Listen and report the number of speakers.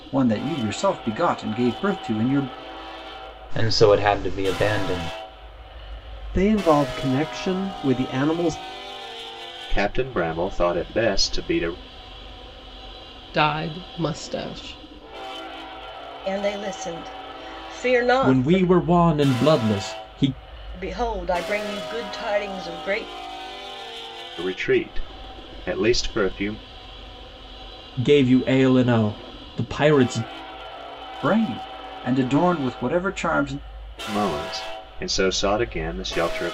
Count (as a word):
seven